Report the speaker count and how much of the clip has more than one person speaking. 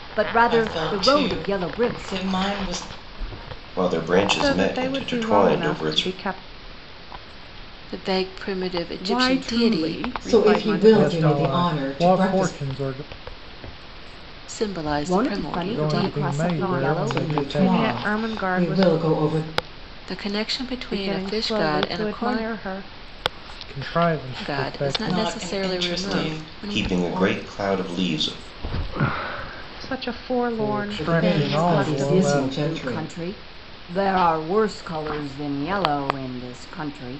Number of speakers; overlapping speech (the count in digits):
8, about 49%